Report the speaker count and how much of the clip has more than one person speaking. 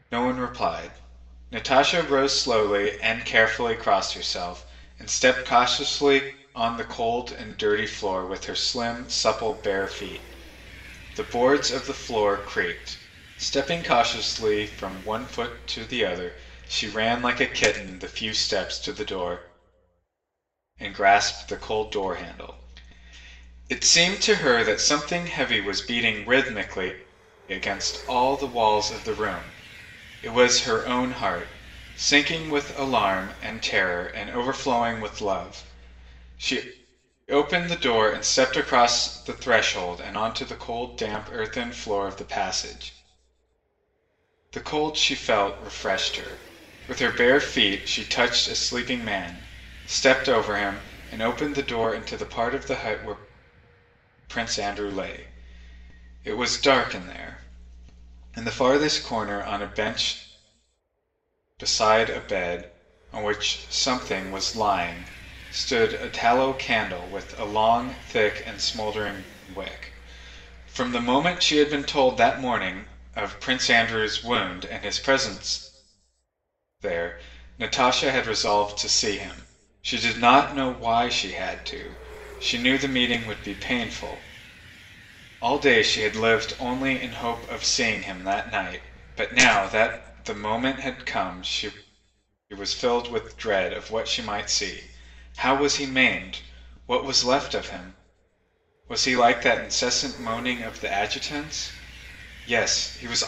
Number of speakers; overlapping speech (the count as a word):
one, no overlap